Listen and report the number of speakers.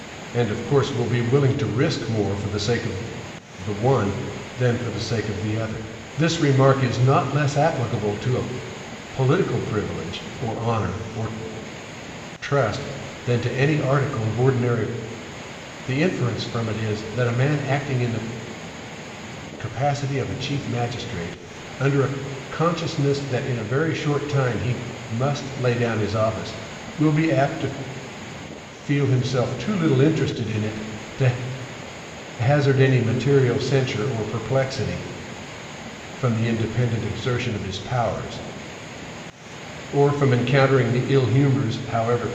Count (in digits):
1